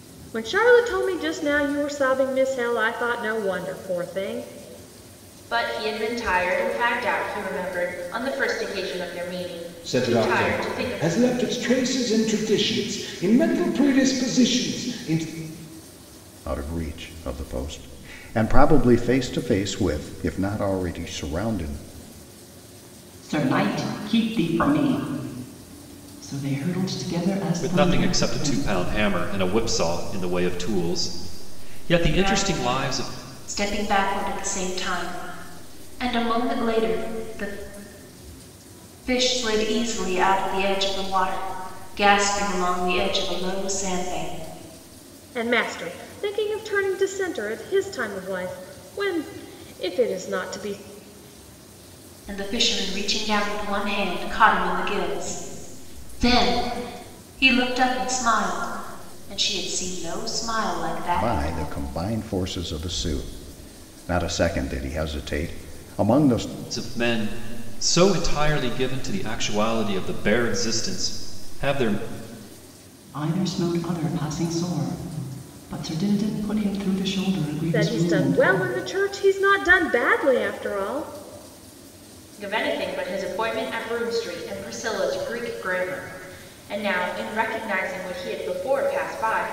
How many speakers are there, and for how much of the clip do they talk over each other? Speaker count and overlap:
7, about 5%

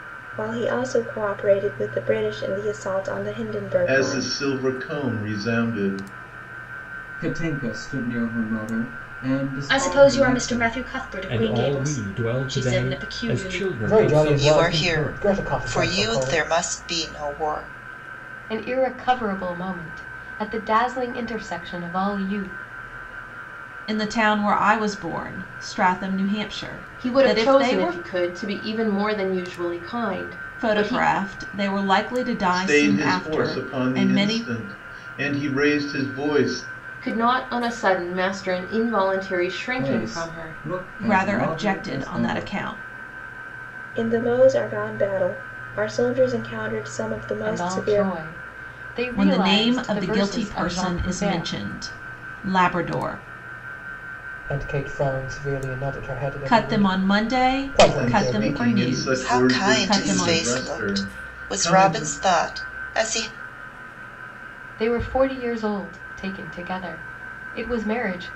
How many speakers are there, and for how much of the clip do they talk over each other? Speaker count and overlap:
10, about 32%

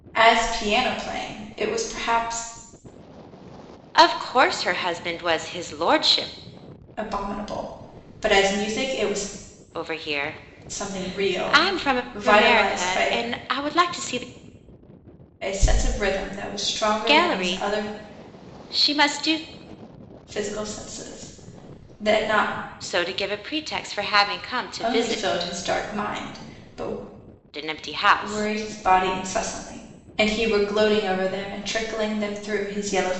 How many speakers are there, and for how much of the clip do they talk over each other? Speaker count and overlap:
2, about 12%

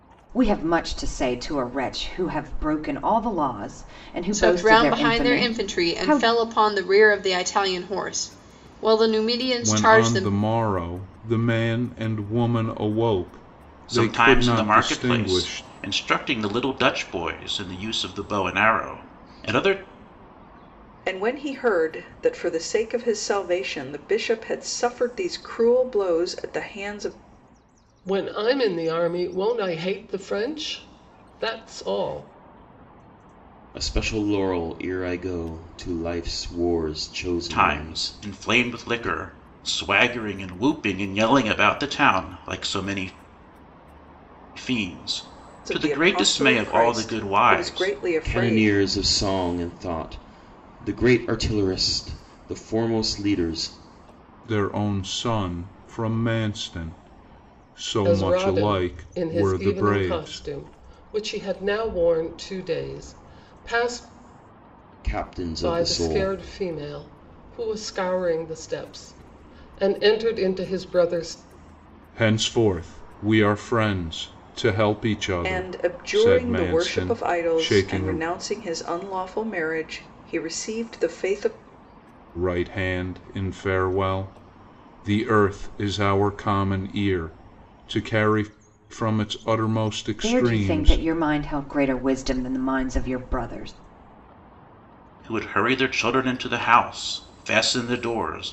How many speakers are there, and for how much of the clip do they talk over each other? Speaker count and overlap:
7, about 16%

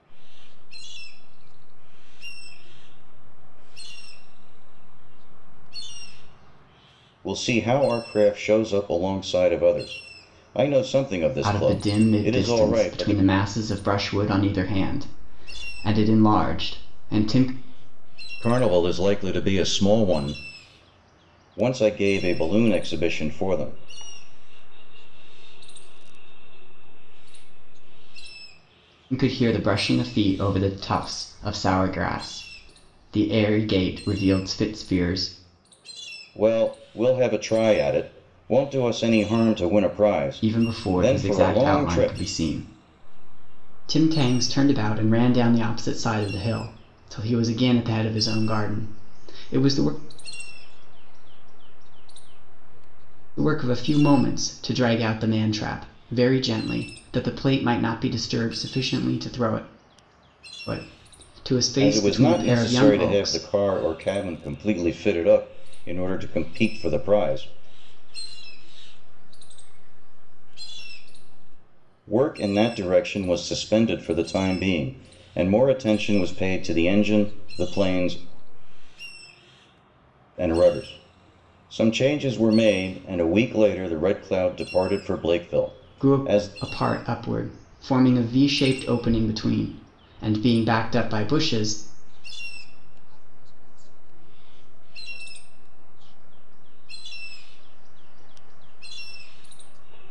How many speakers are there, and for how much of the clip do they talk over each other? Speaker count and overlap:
3, about 23%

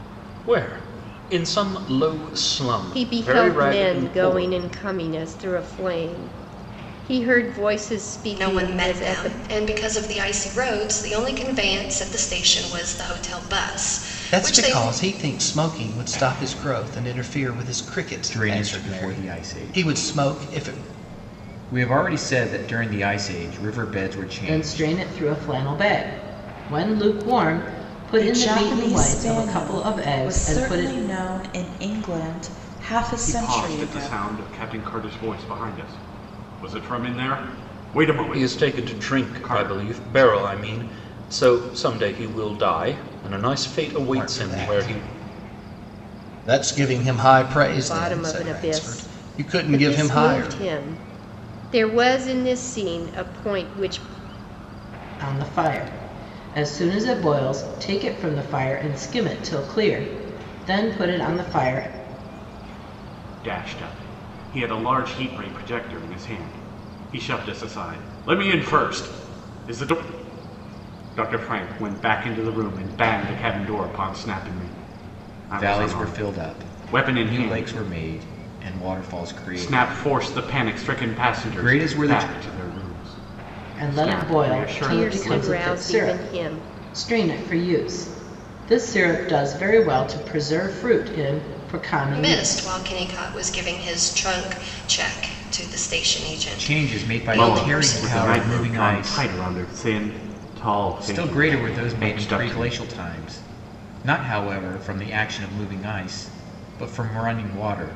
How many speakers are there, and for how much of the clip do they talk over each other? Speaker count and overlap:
8, about 26%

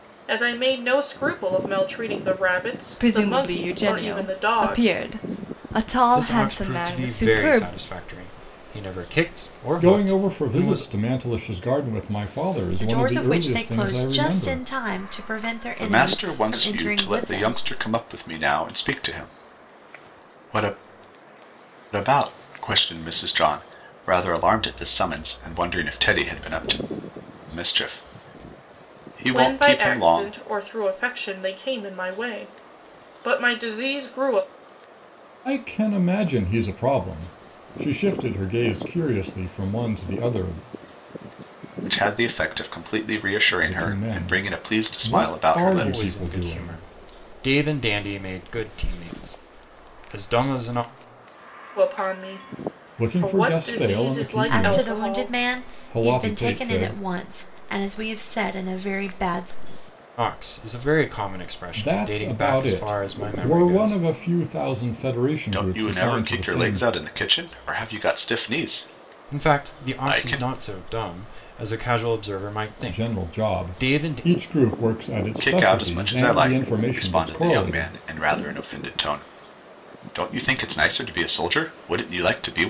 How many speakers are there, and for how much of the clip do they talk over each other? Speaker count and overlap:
6, about 31%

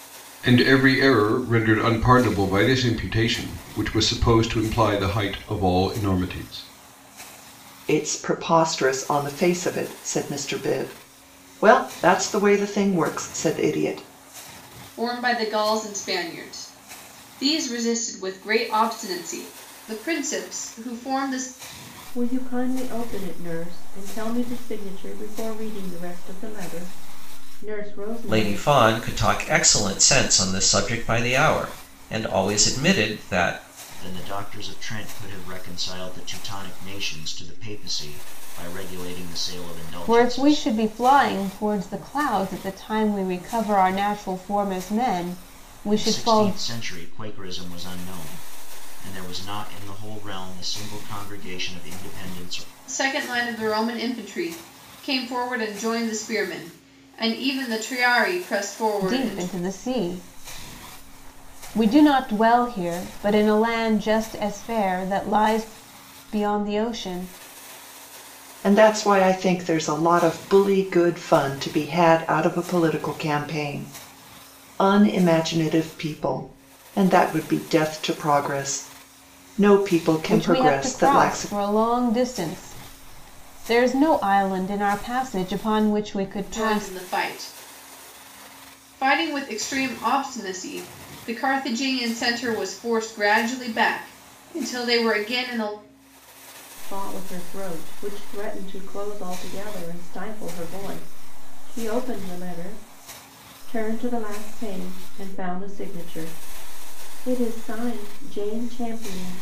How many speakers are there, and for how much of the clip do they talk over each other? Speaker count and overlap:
7, about 4%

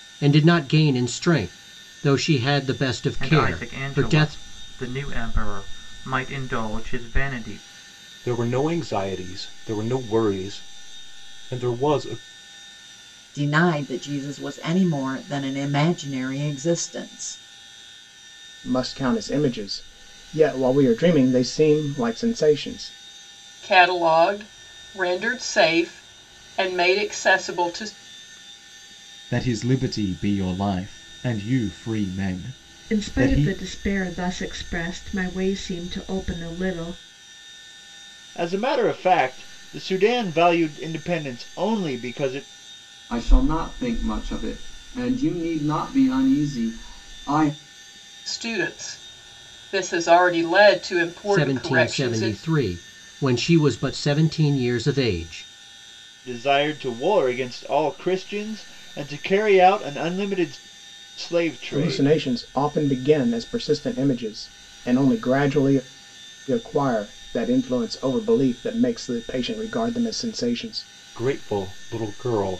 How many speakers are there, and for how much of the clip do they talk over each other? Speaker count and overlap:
10, about 5%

